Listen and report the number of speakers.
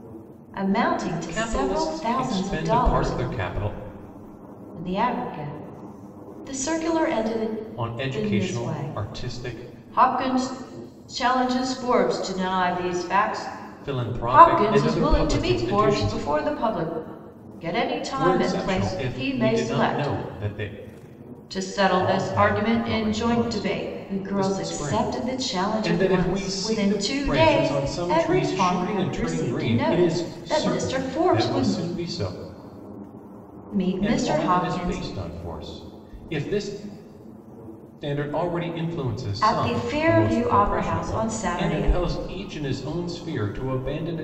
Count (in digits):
2